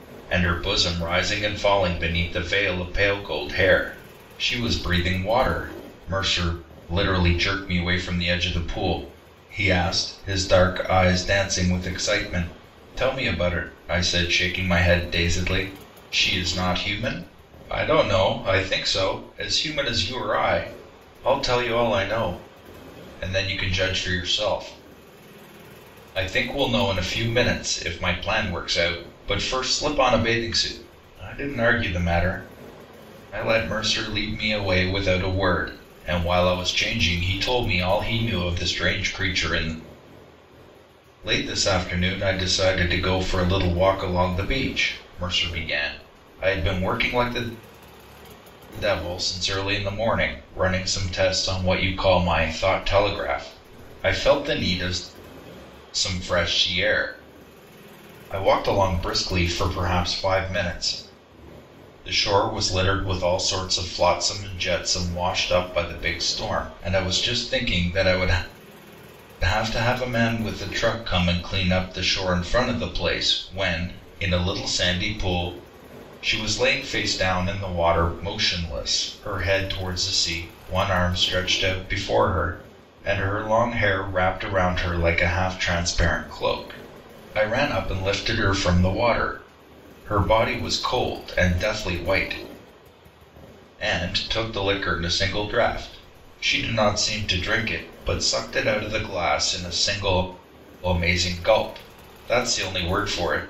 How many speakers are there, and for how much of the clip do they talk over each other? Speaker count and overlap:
1, no overlap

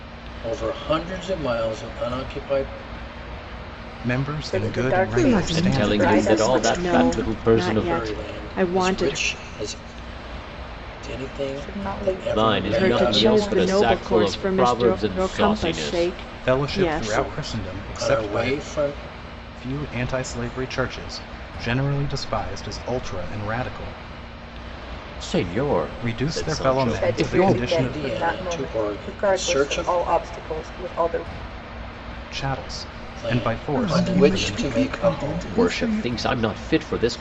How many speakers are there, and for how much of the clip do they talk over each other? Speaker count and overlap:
6, about 49%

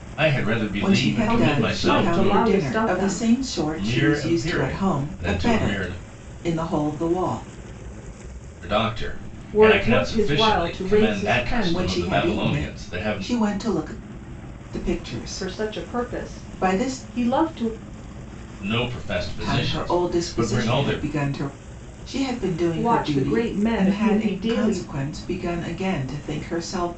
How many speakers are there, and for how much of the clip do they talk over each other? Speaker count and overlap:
3, about 52%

